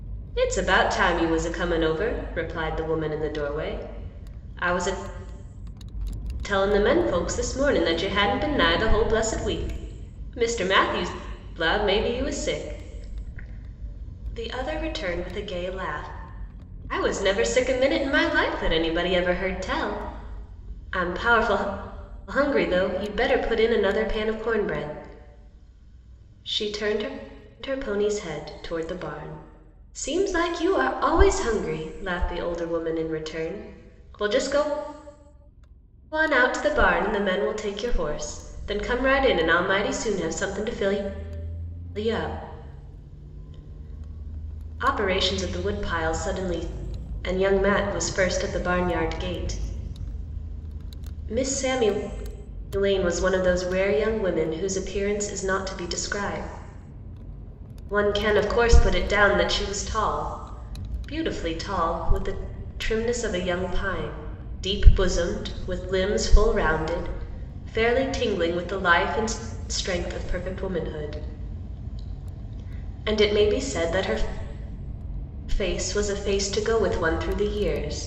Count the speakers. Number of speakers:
1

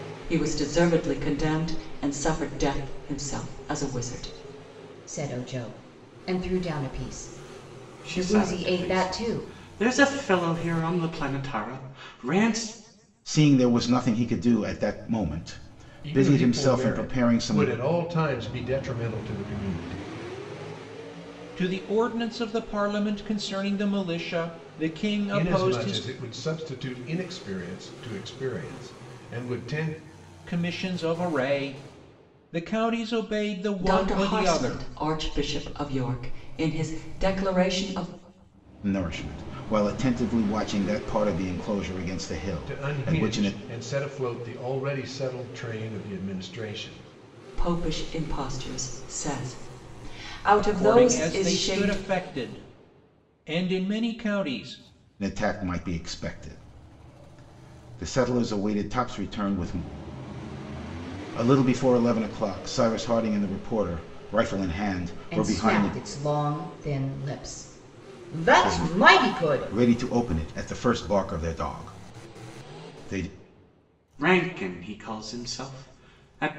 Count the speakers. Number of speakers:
6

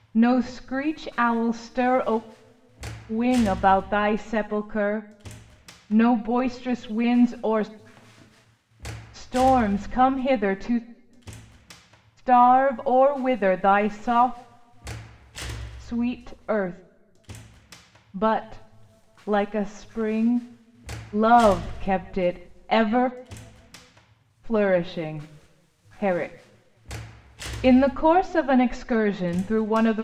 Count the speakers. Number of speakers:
1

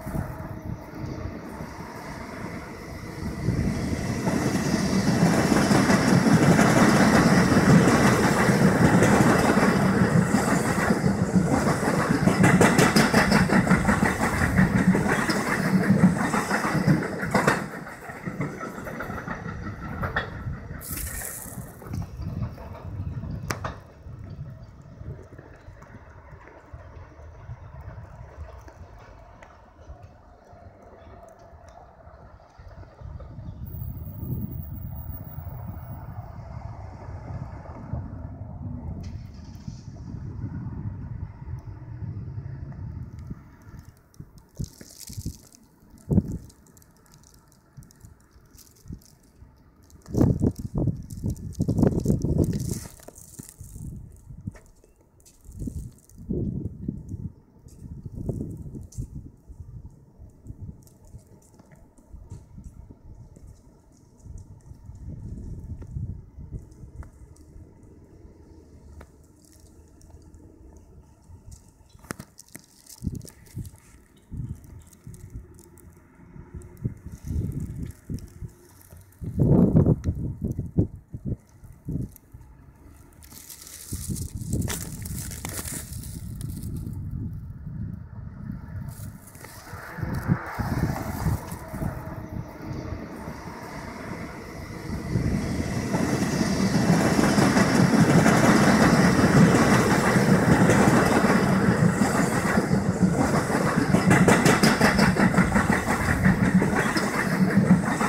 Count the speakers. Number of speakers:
0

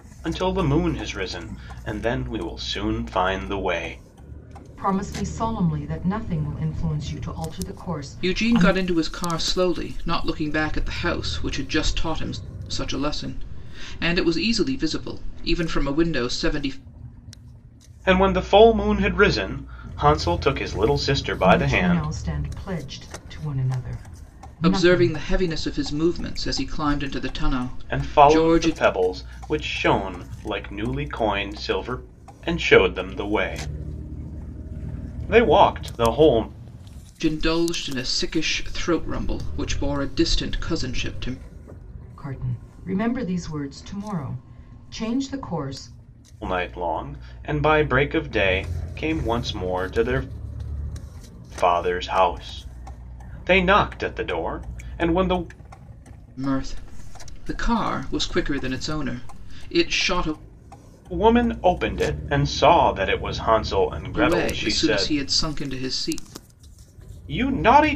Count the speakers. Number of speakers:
3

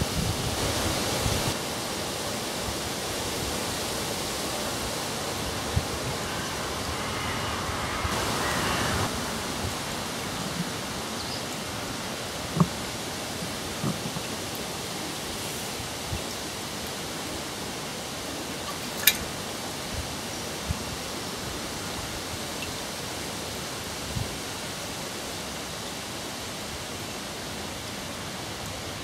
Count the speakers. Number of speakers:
0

